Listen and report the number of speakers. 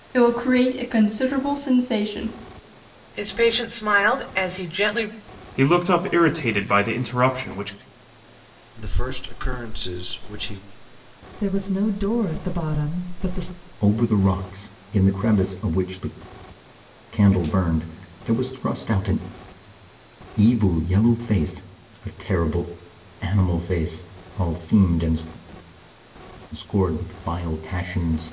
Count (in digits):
6